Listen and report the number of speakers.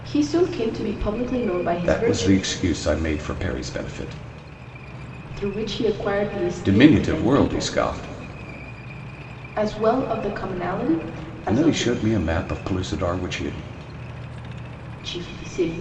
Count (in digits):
2